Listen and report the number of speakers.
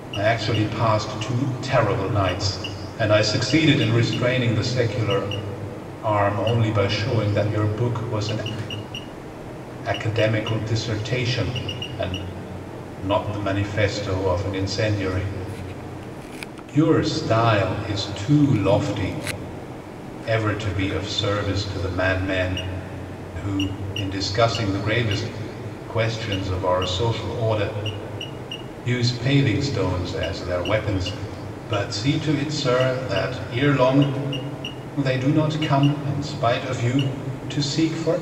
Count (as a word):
one